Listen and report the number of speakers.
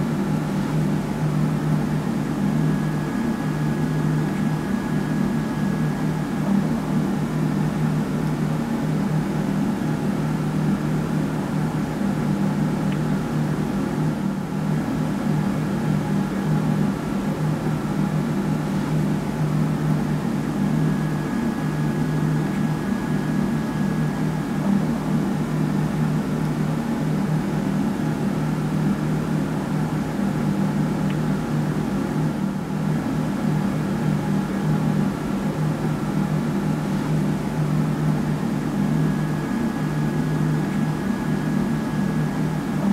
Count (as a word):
zero